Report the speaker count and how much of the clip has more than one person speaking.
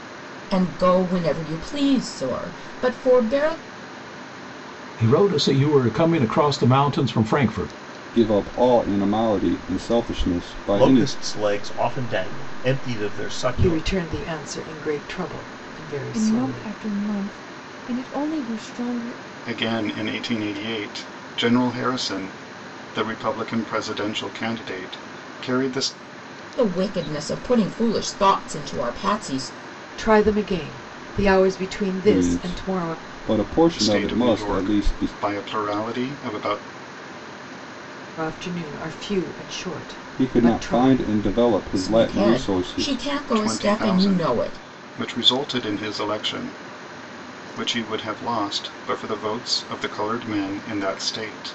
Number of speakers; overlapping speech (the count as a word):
seven, about 14%